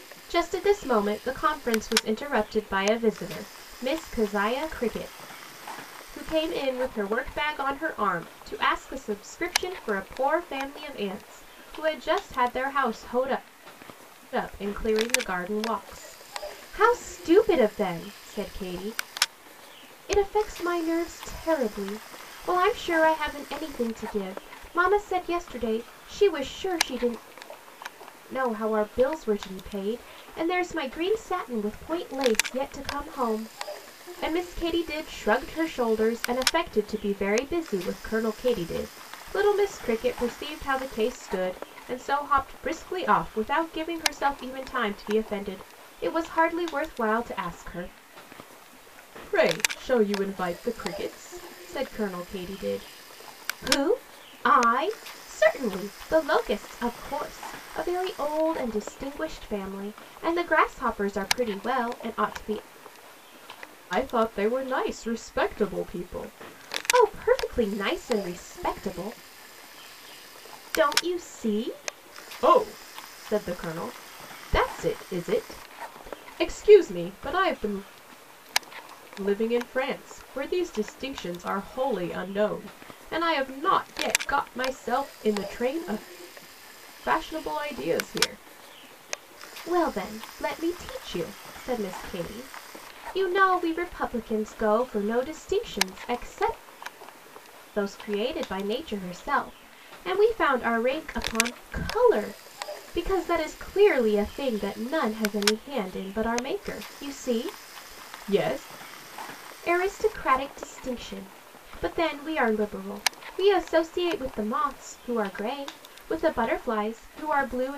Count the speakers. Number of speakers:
1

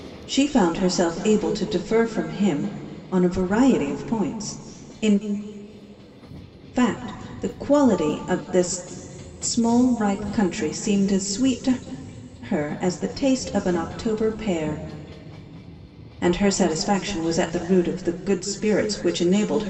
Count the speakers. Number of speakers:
1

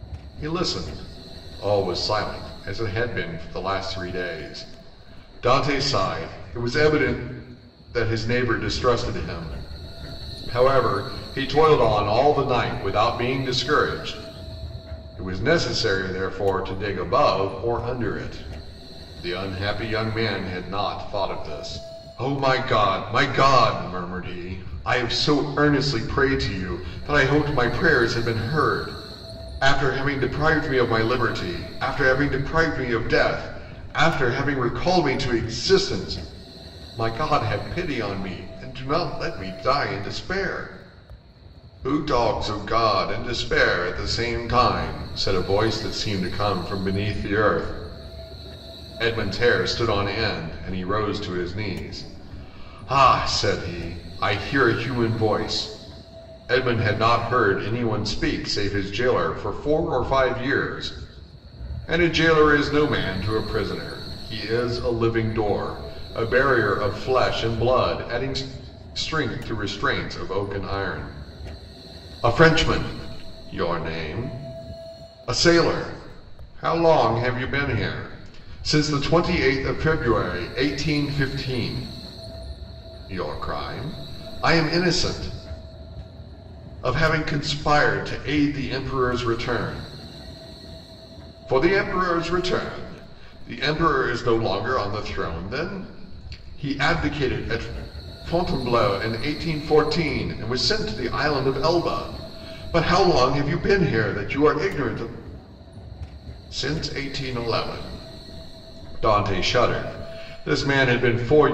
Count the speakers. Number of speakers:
1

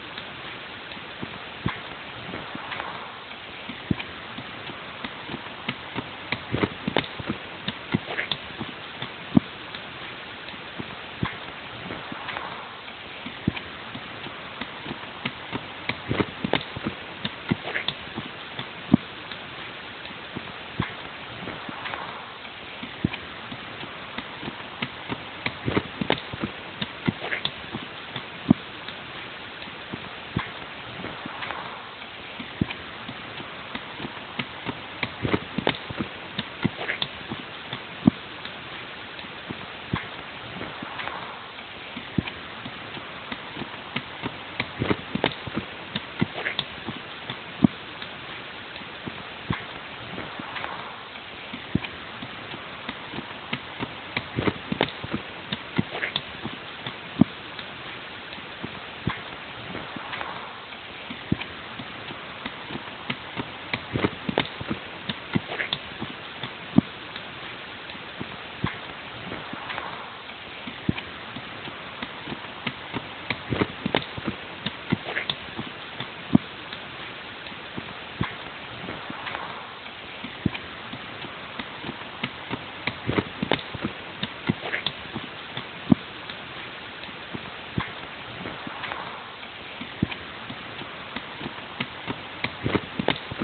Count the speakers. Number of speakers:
0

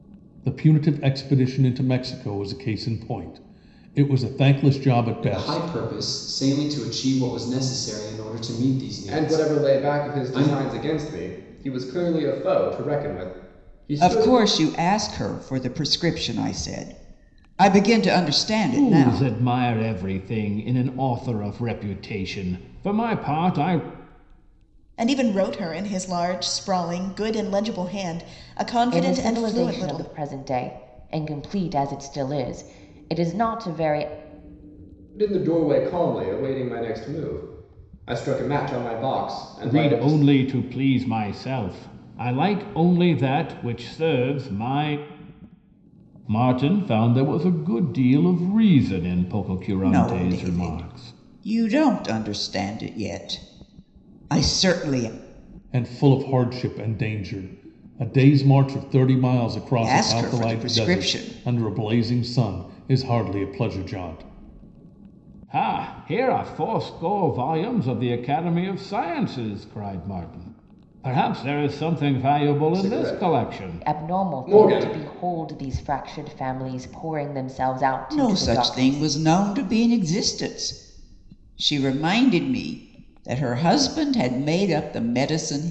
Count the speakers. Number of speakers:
7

